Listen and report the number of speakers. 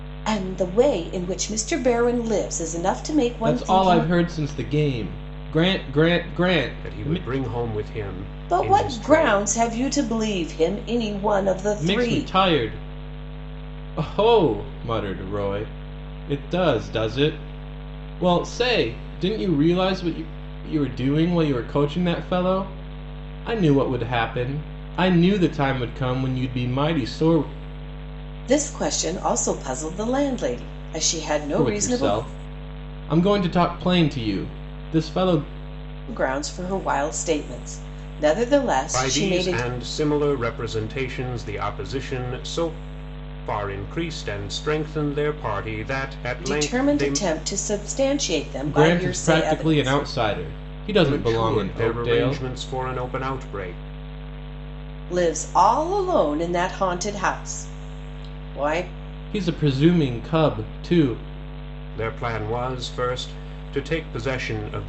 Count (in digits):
3